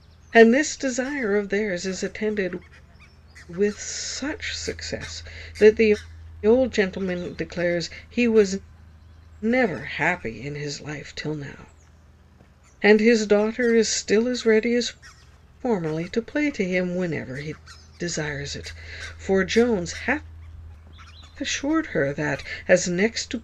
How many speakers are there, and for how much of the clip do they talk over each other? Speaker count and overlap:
1, no overlap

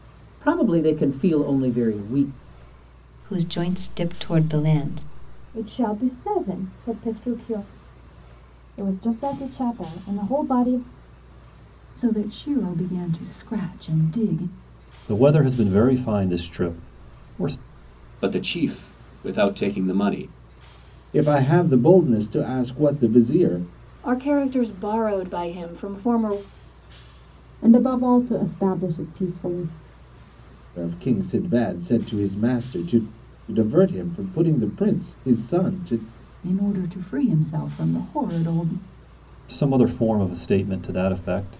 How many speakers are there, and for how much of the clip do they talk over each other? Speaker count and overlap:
10, no overlap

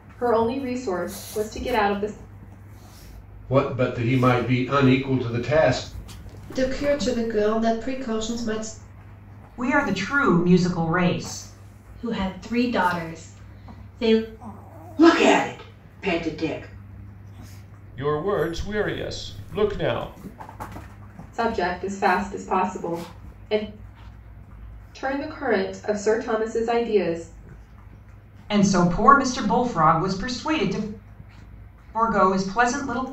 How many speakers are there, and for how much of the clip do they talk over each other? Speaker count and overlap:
7, no overlap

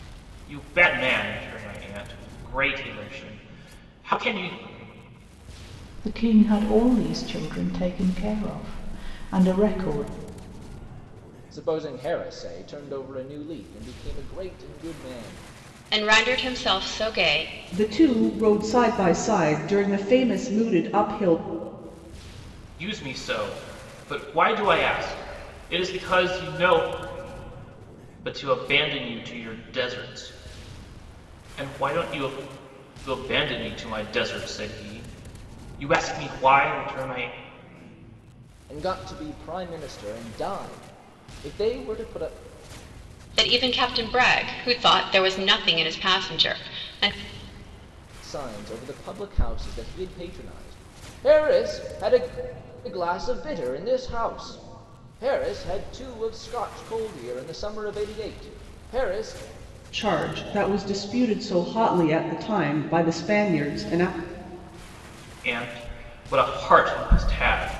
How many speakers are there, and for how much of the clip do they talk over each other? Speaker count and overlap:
5, no overlap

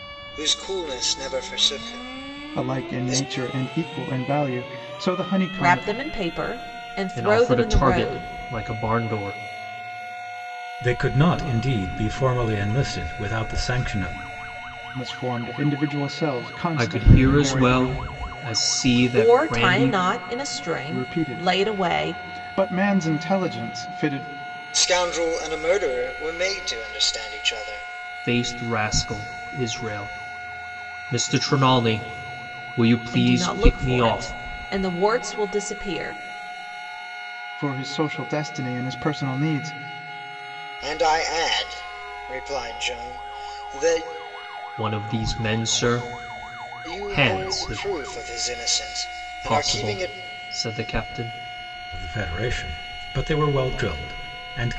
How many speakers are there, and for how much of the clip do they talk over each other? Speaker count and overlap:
5, about 16%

